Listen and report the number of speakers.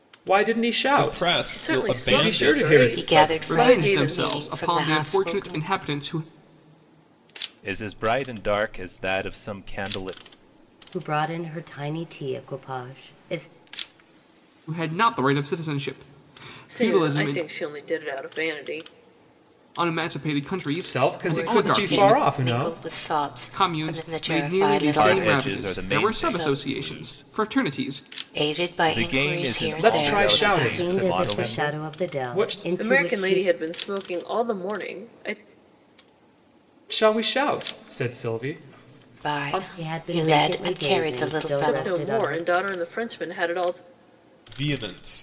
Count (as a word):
seven